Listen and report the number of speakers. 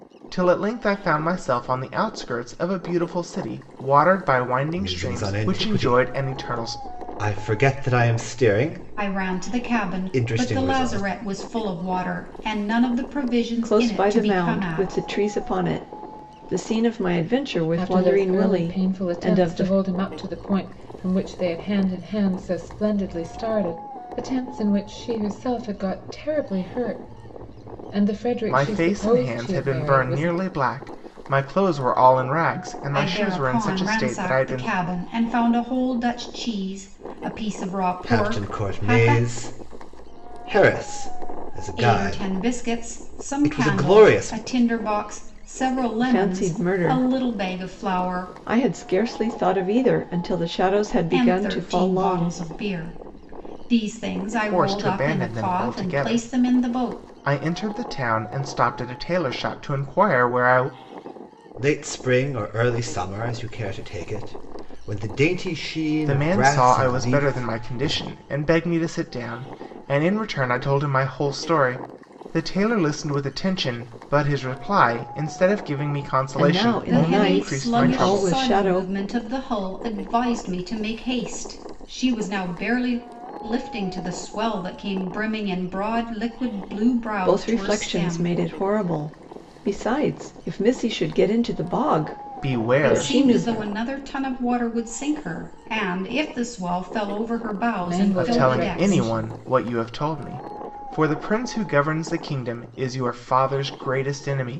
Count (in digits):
5